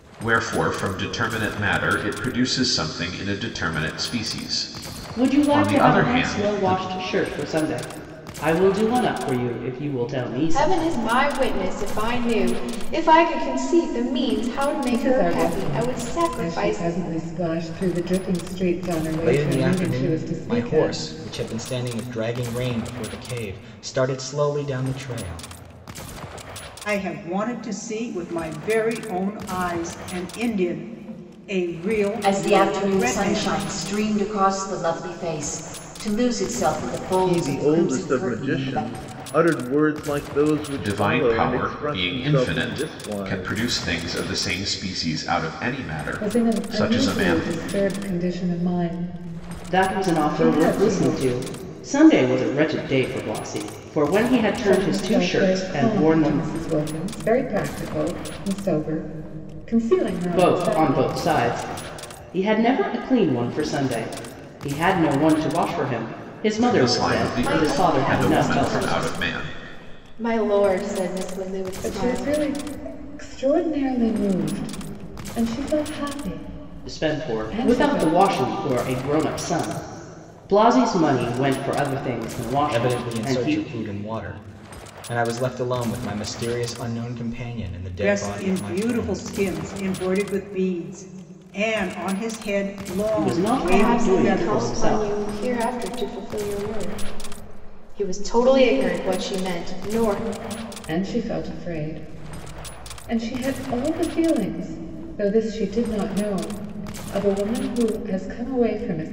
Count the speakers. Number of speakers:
8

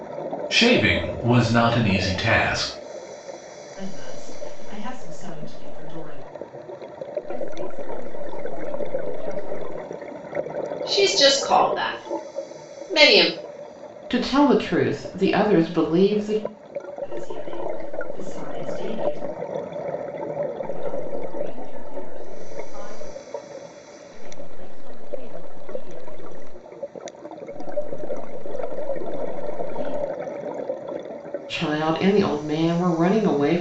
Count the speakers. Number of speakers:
5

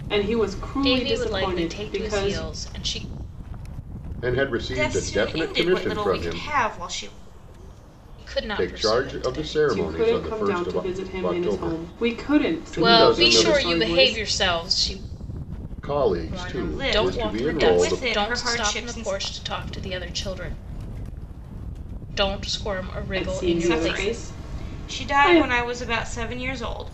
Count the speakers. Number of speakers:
4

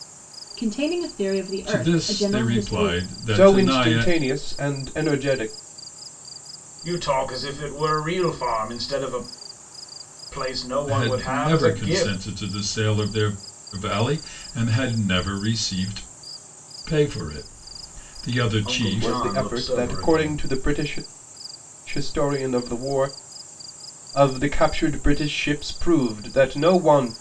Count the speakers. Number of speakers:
4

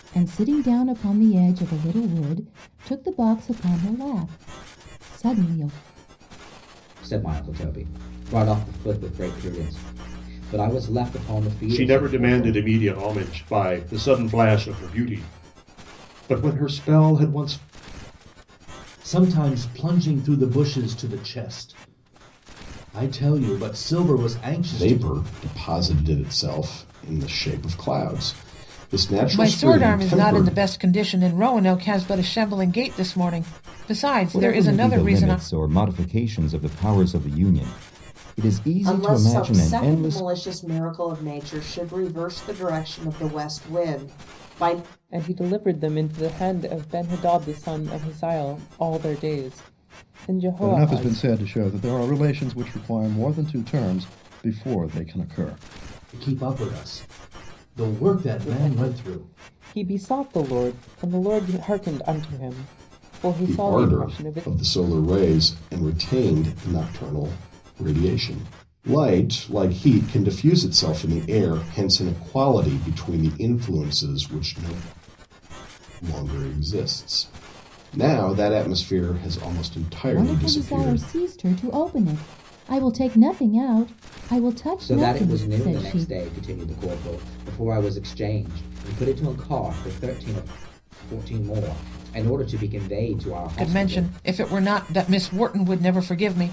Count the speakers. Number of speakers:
10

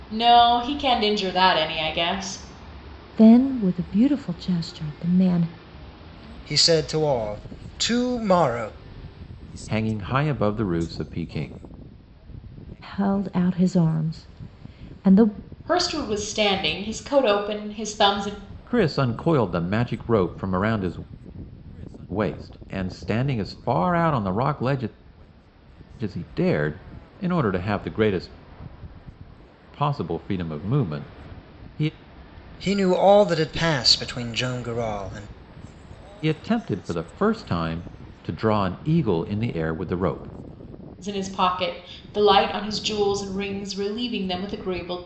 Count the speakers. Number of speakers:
4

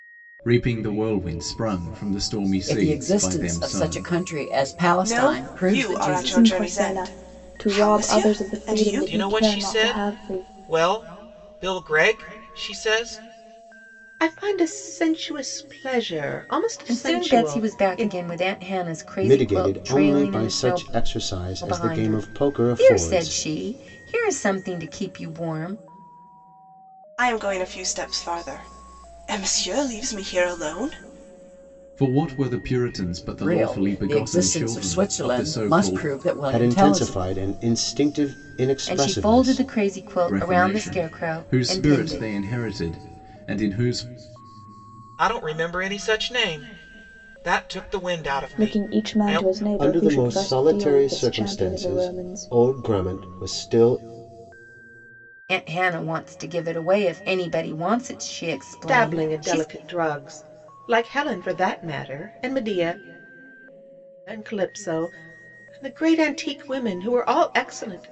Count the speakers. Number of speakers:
8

